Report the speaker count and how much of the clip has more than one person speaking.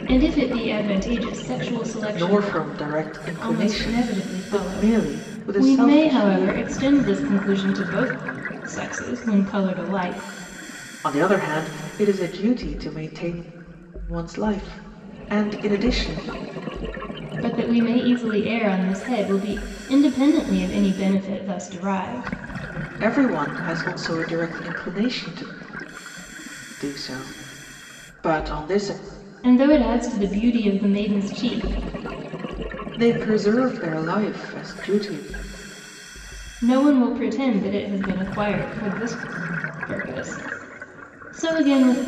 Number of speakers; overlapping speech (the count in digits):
2, about 9%